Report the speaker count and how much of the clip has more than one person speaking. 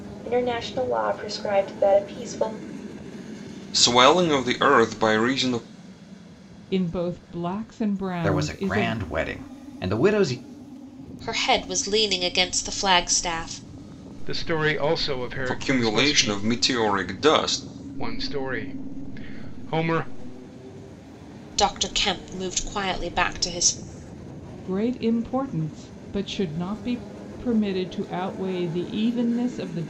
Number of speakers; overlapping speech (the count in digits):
6, about 6%